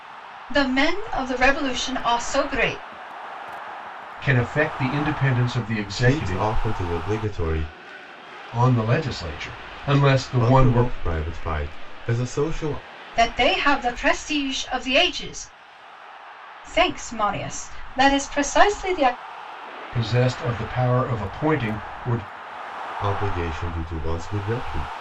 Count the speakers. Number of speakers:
3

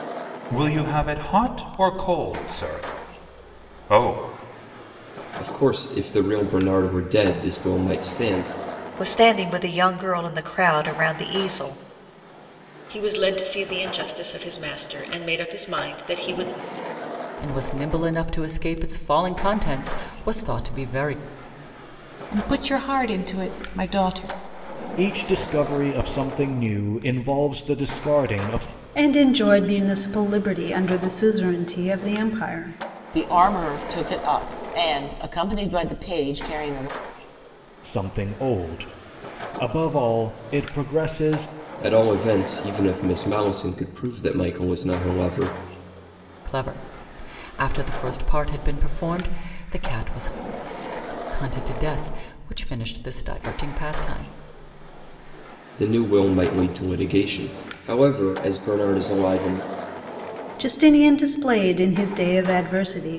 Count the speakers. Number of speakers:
9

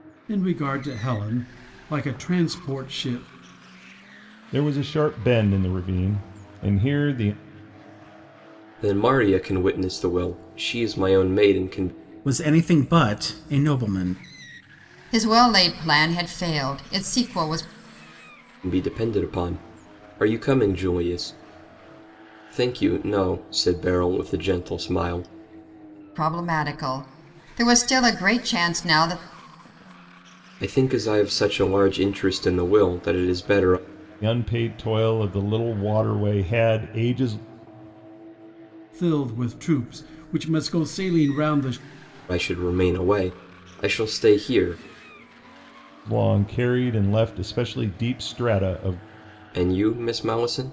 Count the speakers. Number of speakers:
5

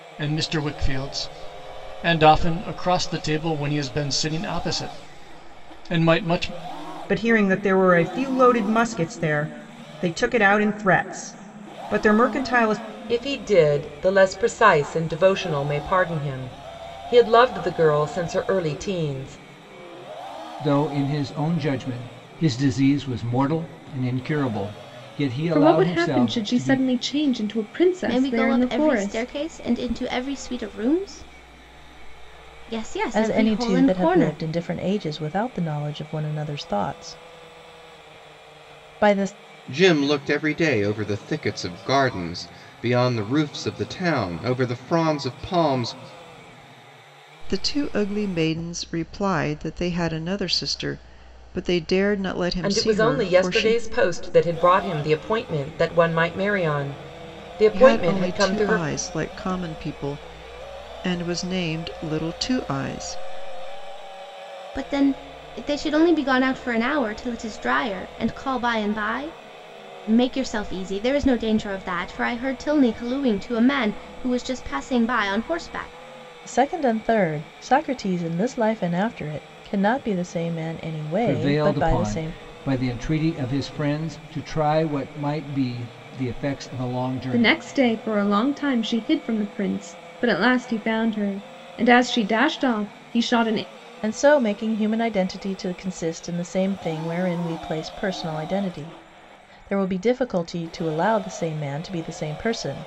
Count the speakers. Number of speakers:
9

